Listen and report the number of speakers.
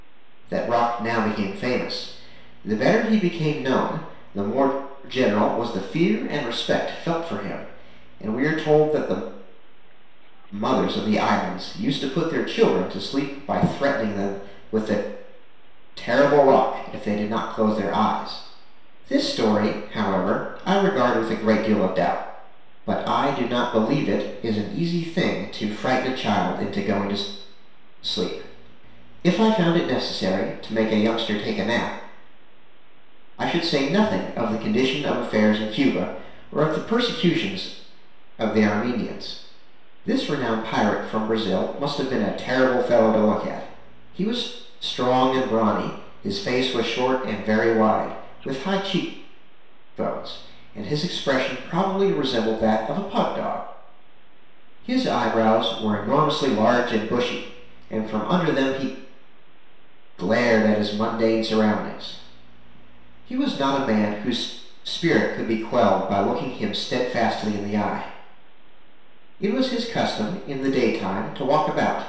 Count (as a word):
one